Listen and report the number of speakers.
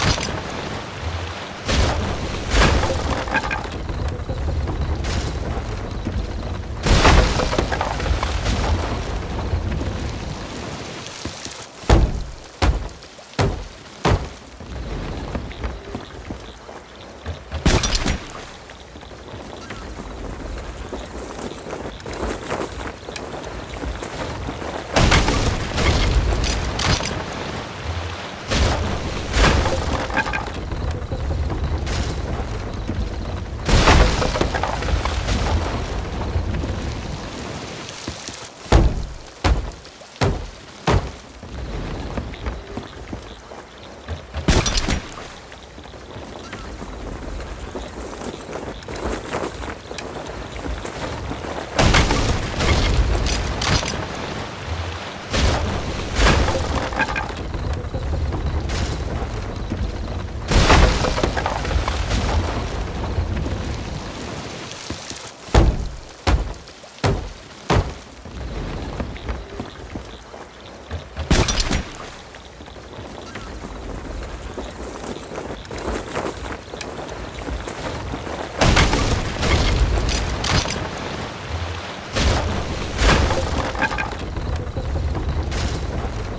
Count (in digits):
0